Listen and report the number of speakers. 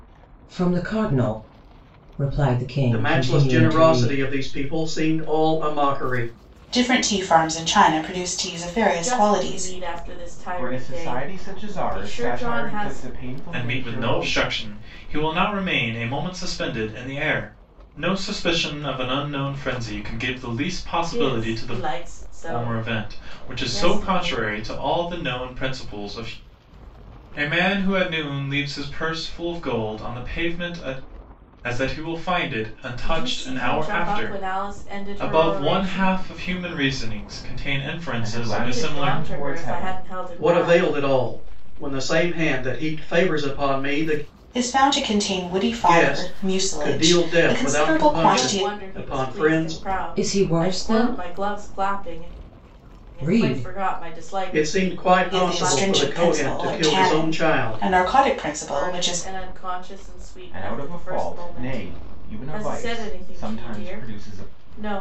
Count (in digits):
6